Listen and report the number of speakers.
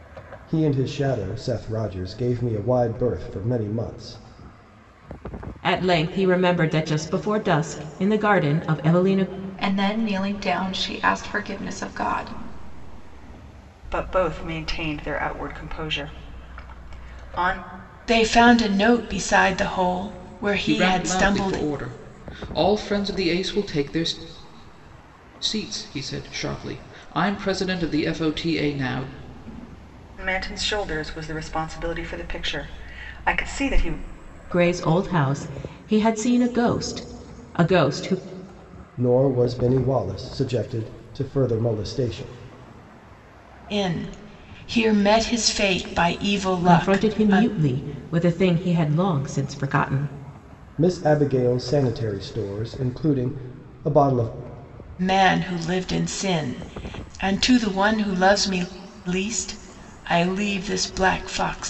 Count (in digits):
6